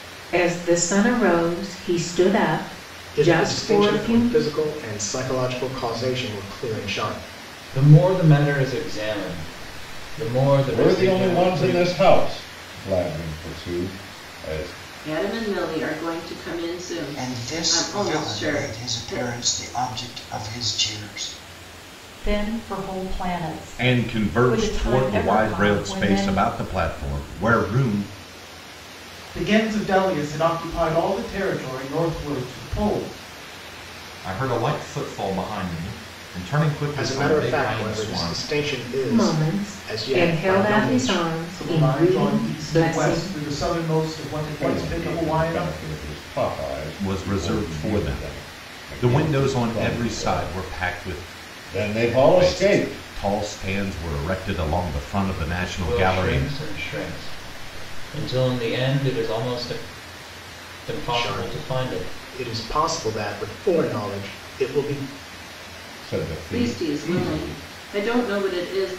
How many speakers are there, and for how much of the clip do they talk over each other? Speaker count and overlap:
ten, about 31%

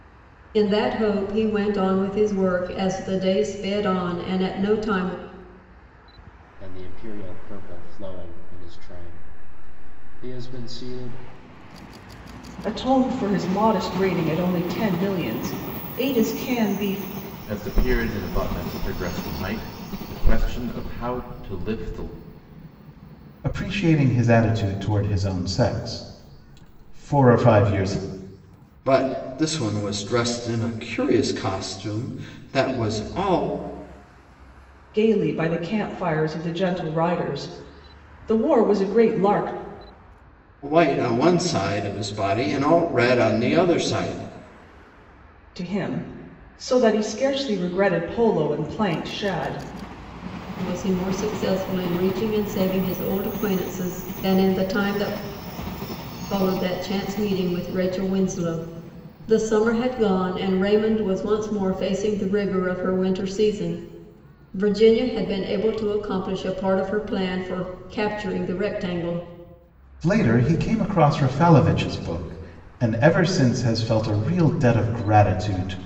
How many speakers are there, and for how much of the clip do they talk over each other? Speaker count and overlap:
six, no overlap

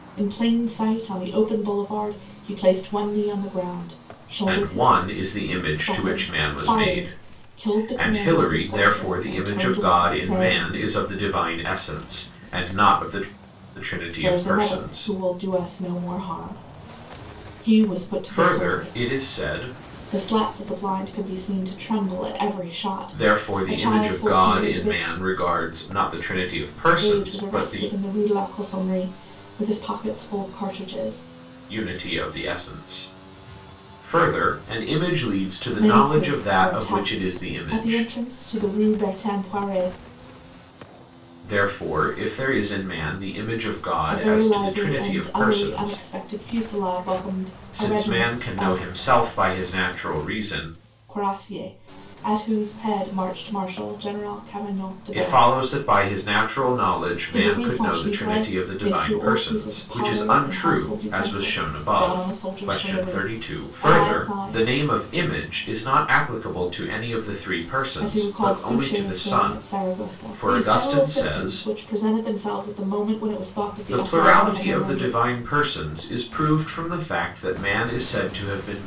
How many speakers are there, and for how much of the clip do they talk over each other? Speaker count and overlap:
two, about 36%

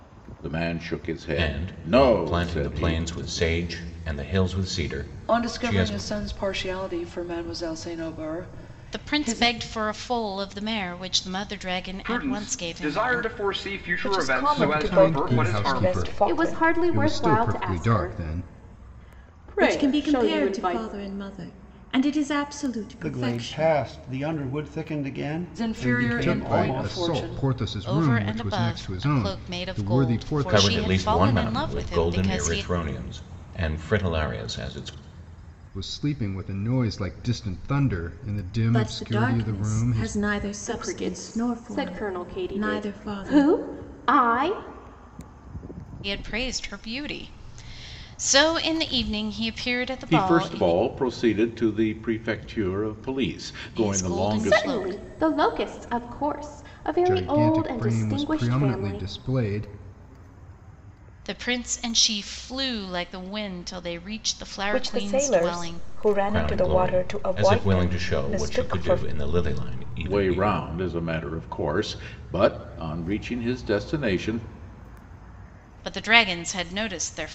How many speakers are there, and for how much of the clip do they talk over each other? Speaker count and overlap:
ten, about 40%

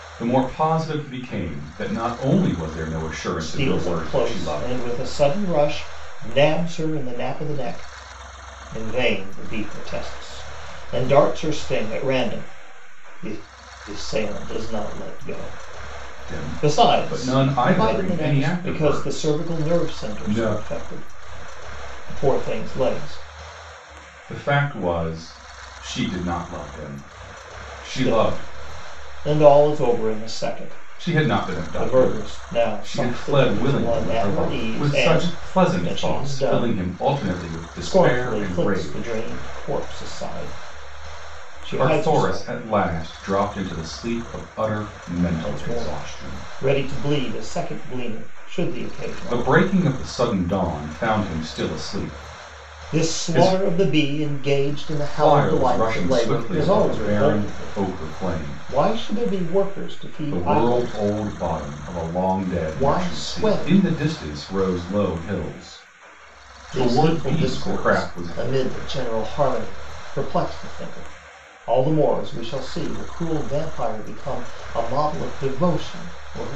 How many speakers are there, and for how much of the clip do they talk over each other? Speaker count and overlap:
two, about 31%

